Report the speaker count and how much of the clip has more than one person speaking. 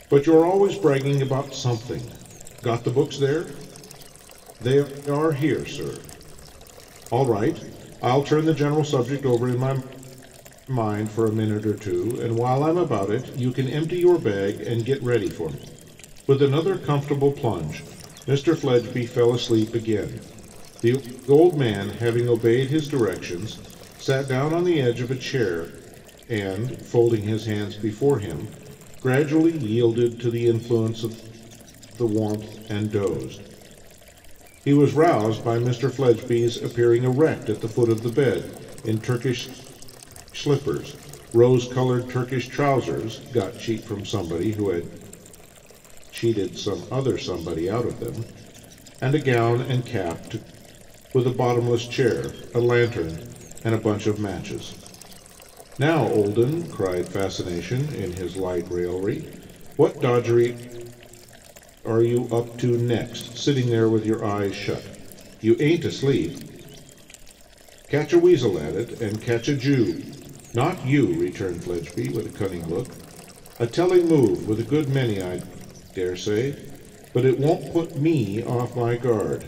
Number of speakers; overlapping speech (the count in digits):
1, no overlap